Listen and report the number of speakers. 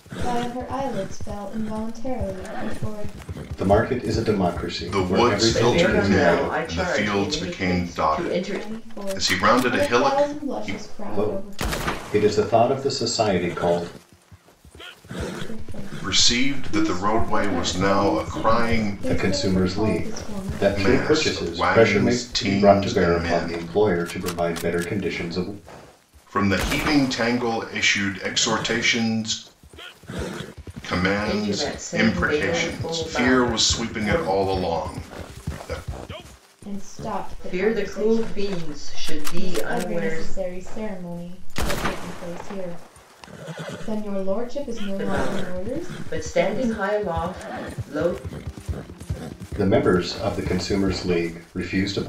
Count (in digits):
4